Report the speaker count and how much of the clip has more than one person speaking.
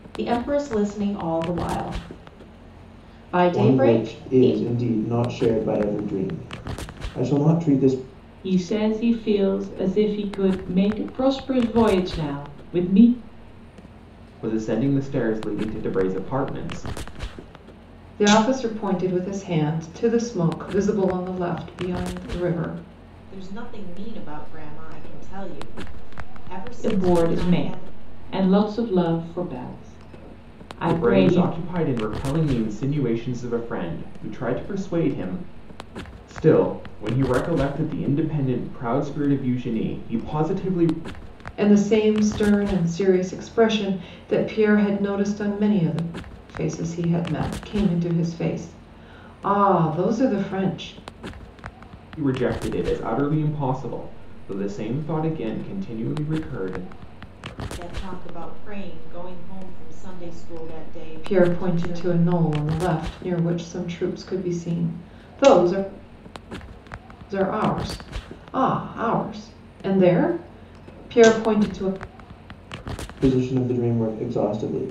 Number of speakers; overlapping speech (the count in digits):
6, about 5%